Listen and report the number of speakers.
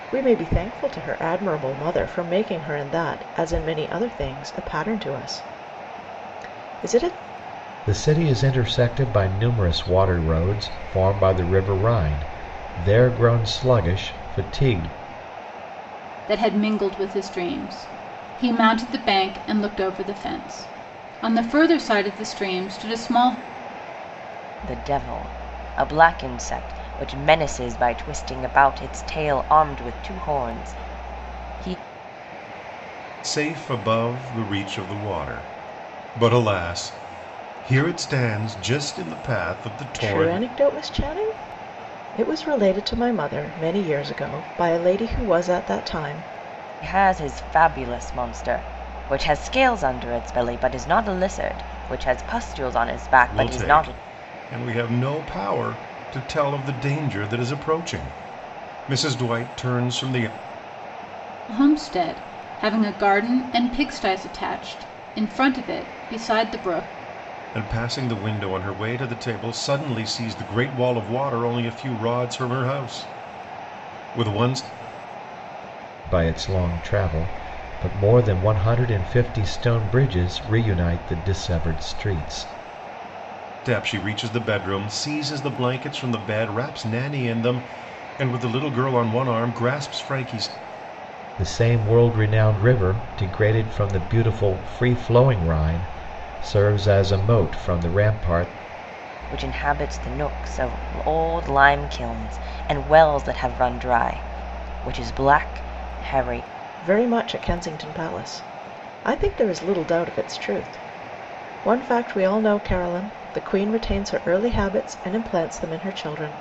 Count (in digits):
5